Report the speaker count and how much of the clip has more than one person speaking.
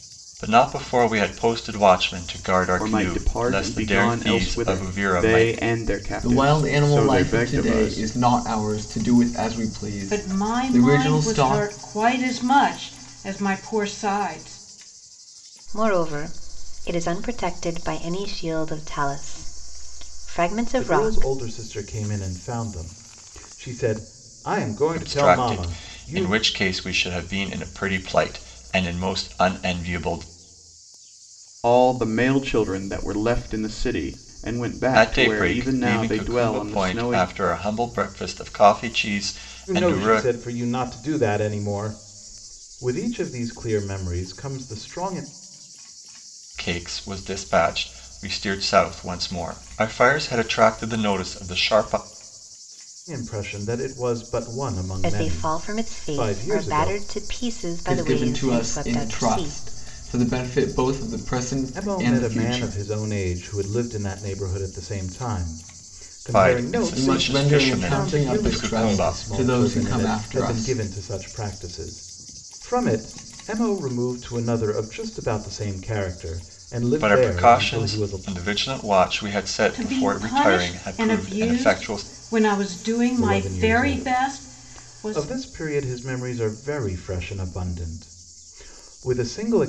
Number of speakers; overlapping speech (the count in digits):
6, about 29%